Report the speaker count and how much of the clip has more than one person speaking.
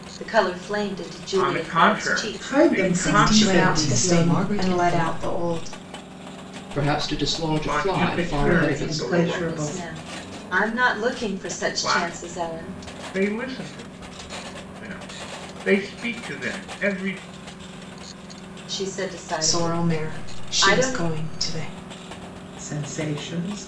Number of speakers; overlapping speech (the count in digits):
6, about 38%